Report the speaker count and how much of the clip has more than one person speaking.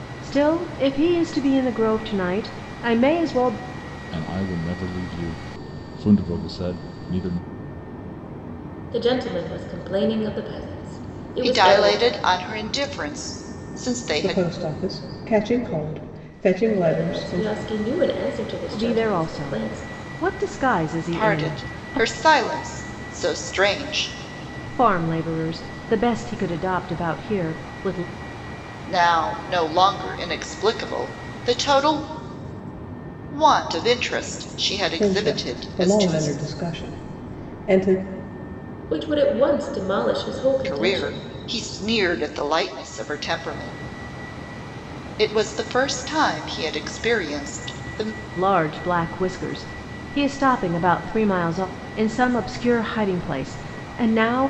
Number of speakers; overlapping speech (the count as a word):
five, about 11%